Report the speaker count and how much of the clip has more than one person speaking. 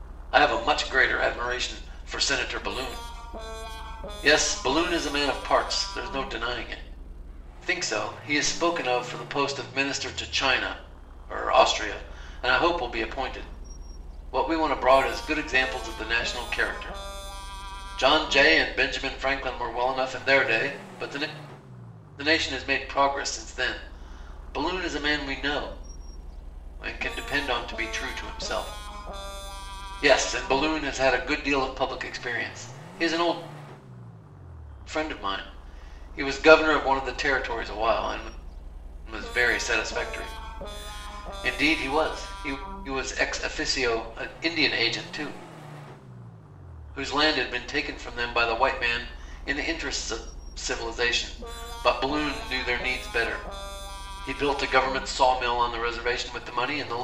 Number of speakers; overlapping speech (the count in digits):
1, no overlap